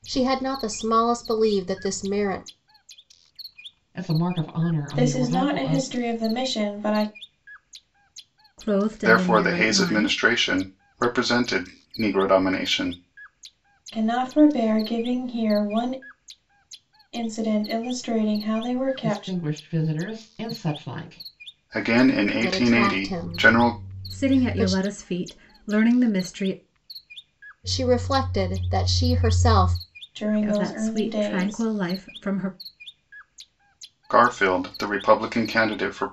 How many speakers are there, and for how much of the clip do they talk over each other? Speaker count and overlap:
5, about 17%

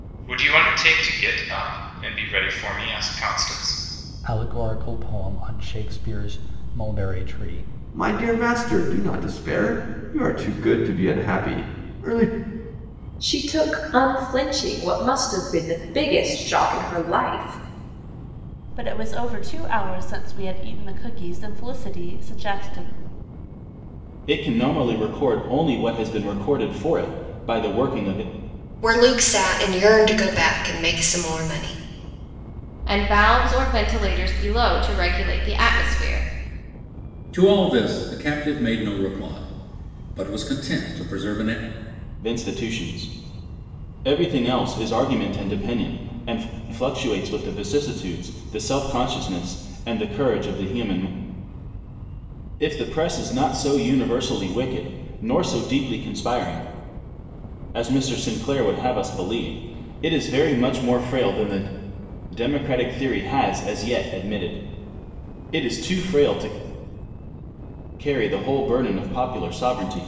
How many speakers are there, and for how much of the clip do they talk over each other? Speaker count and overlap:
9, no overlap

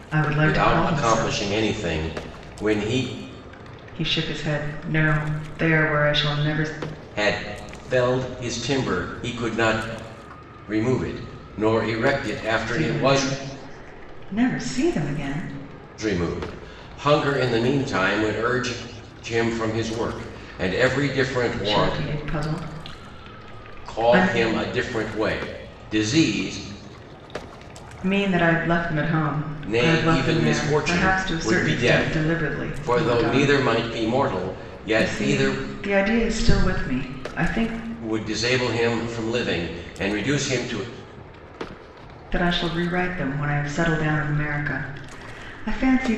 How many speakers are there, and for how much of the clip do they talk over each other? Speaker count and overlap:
2, about 14%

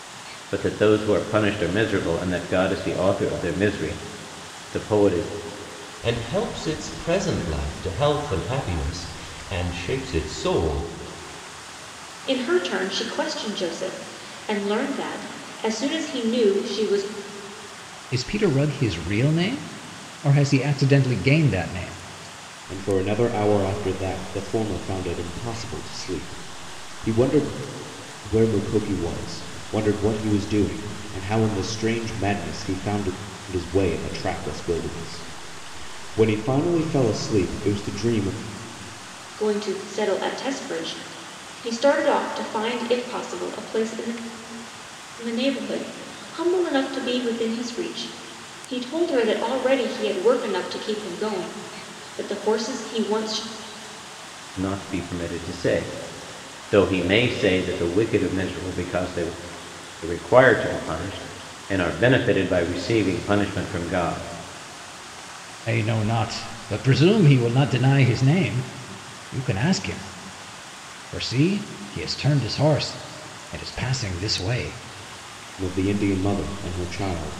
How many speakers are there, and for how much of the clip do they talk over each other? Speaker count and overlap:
5, no overlap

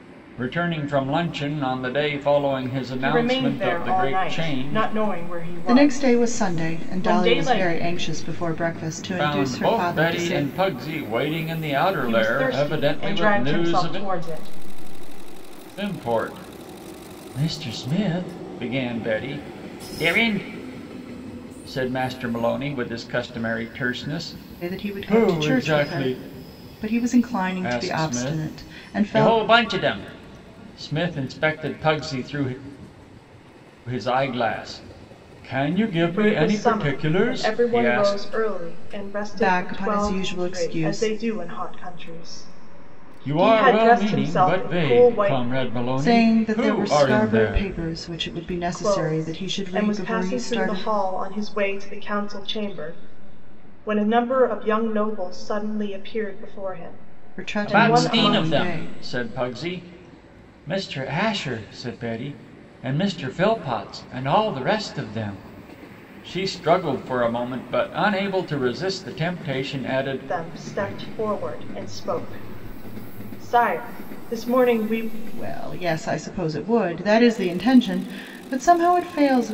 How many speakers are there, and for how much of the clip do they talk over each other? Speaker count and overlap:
3, about 30%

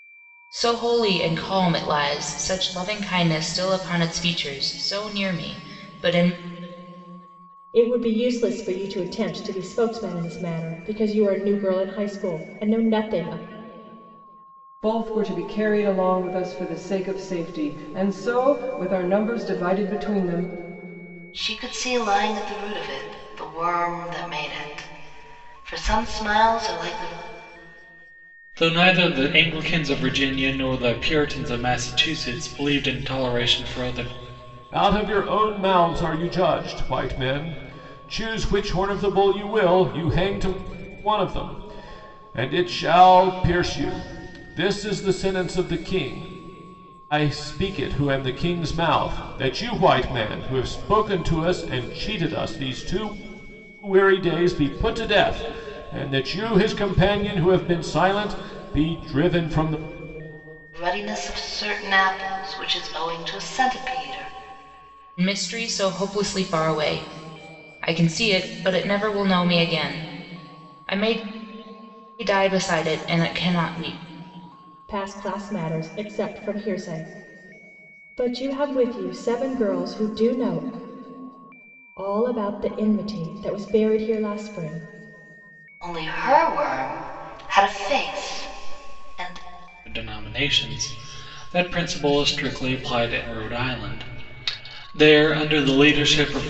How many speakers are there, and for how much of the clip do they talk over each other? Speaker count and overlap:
6, no overlap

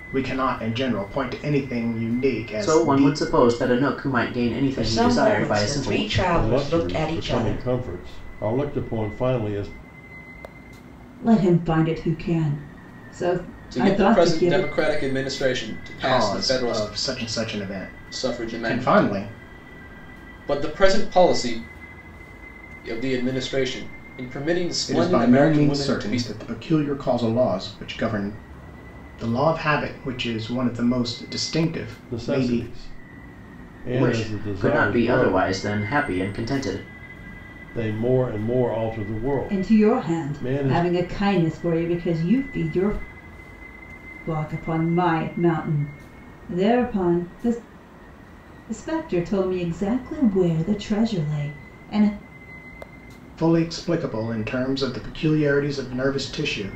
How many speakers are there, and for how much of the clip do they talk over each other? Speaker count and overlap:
6, about 20%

